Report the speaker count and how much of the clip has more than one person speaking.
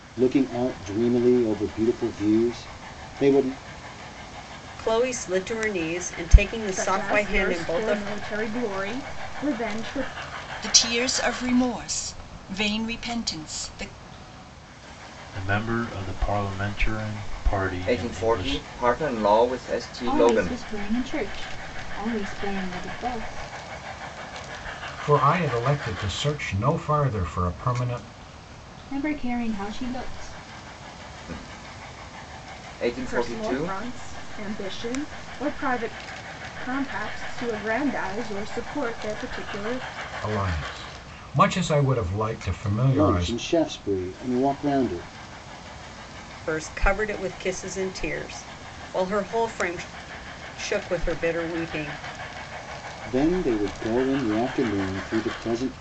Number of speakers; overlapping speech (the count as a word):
eight, about 7%